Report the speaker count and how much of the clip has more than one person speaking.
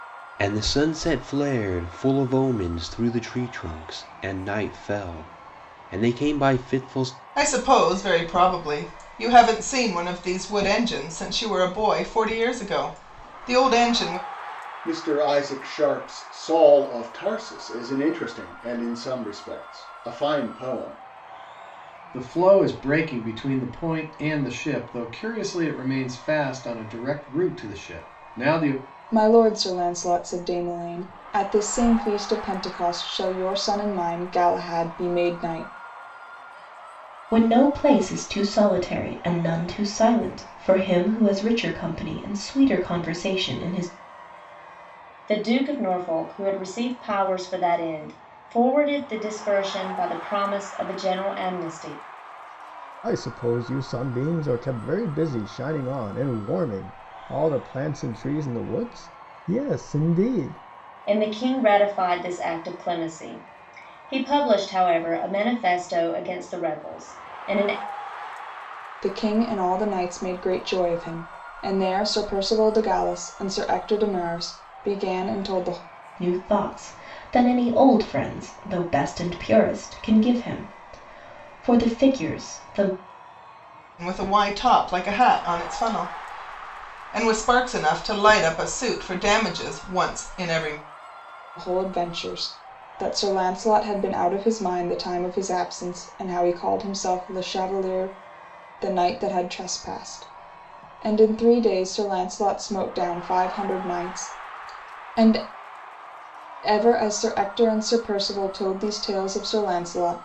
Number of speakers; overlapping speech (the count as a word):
eight, no overlap